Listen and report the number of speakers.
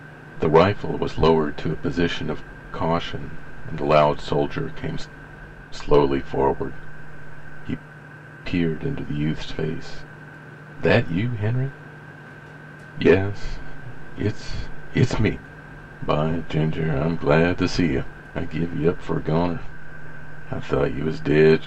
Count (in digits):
1